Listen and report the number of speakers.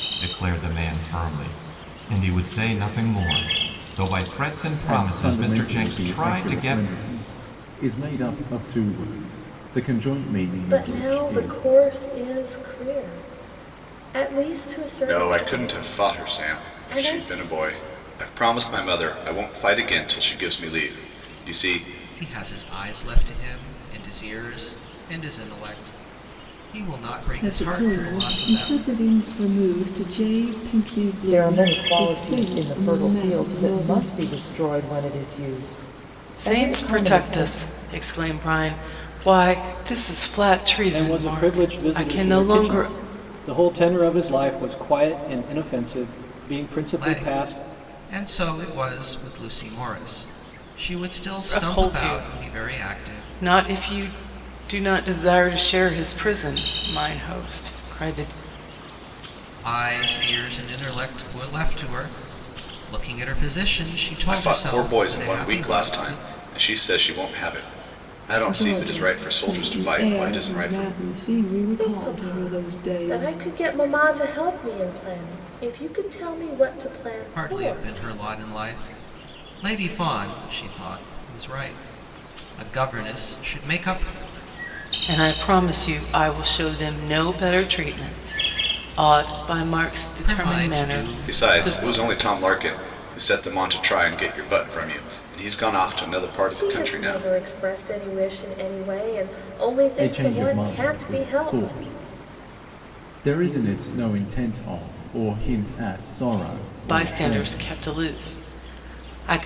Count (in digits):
9